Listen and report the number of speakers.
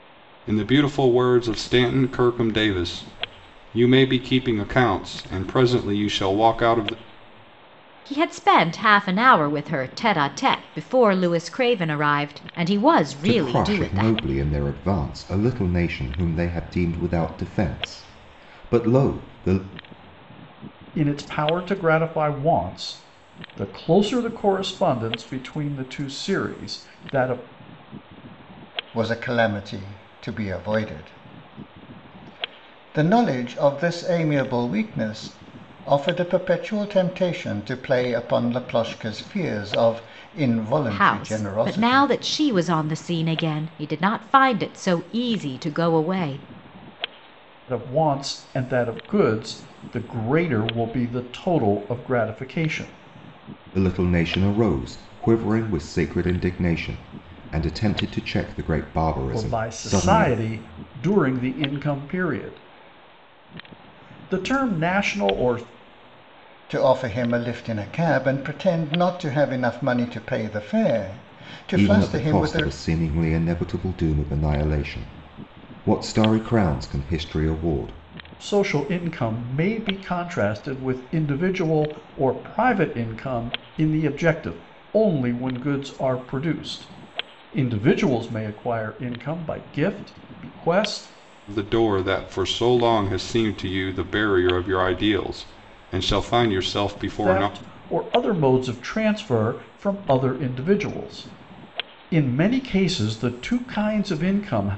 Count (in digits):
5